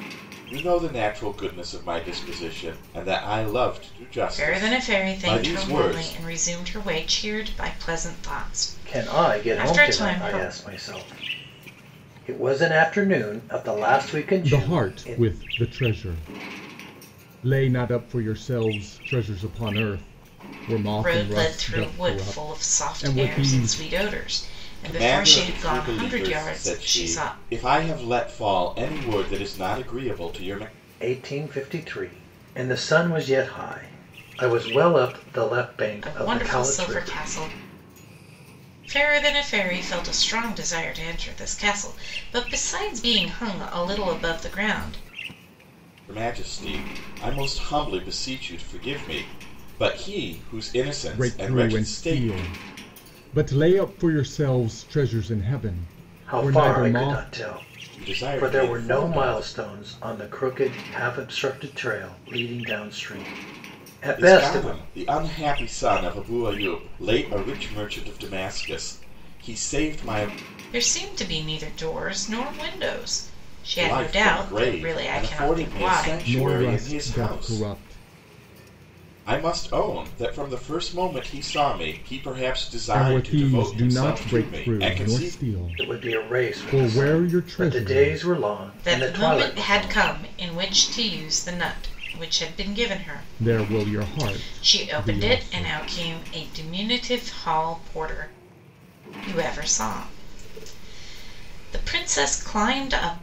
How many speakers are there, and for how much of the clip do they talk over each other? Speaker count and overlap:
4, about 27%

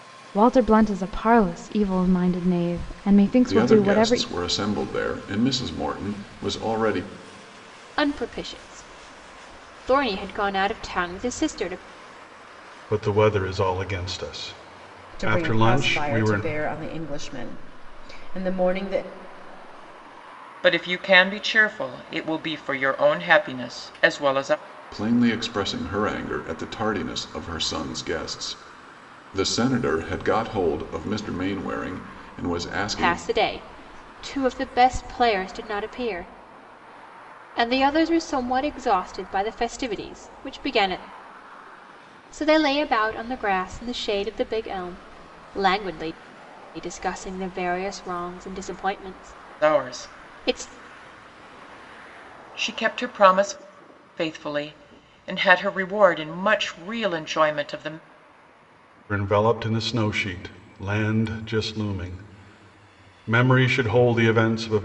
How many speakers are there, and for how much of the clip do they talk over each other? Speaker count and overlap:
6, about 6%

